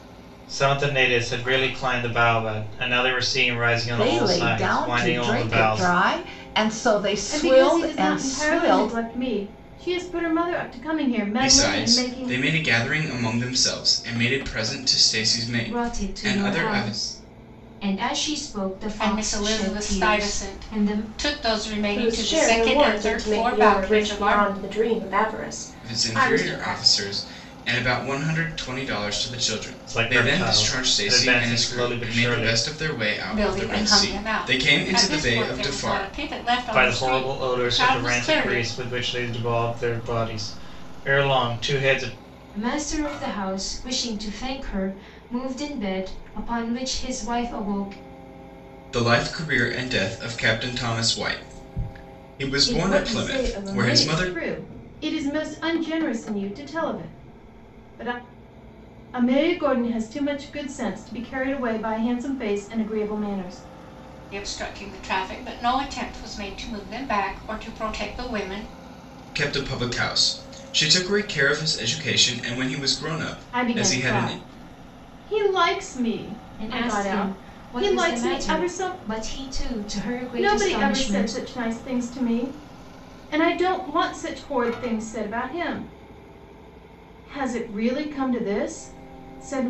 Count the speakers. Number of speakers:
seven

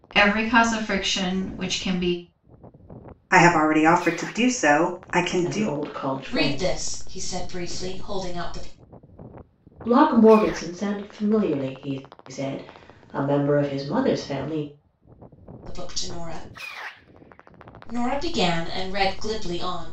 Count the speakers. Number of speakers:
four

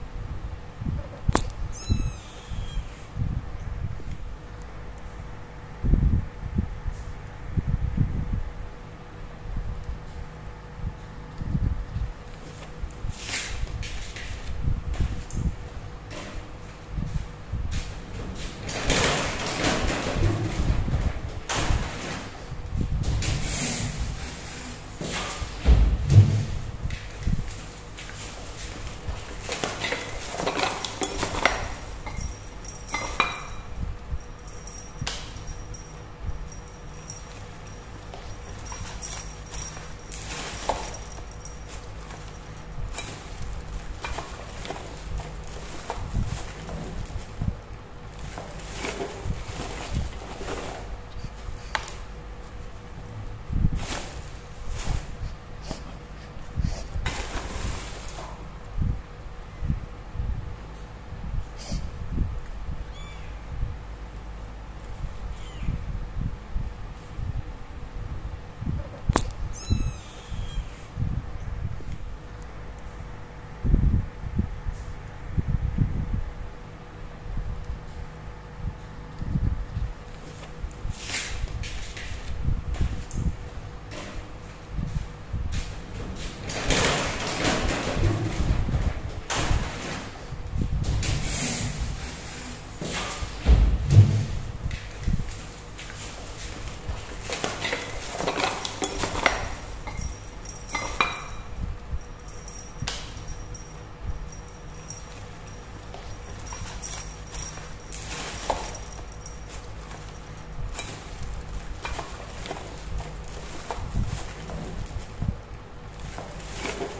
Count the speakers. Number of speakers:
zero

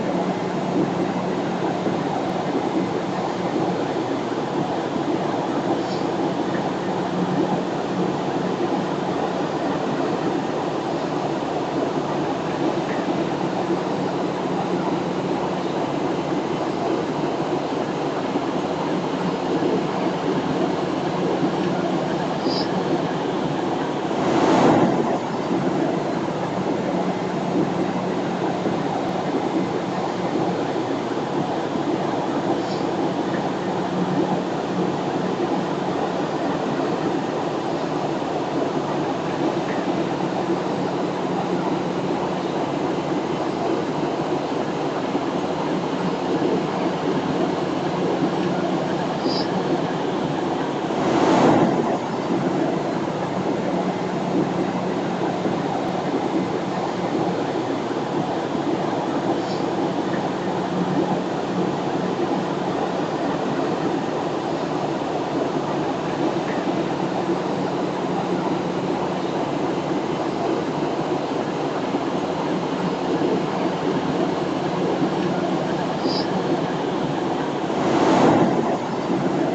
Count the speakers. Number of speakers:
zero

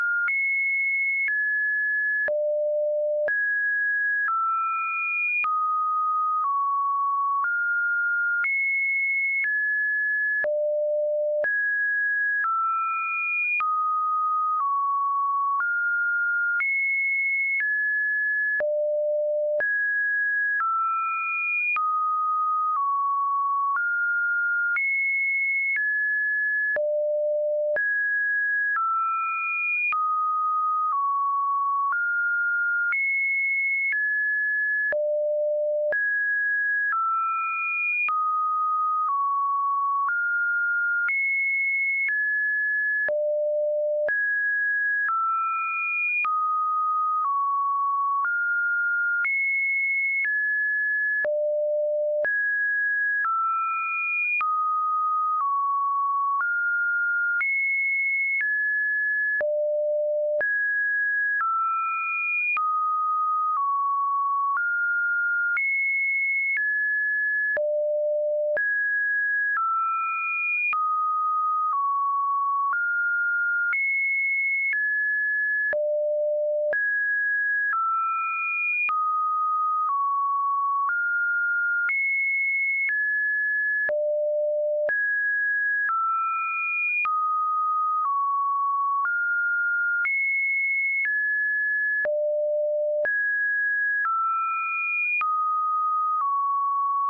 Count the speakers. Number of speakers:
zero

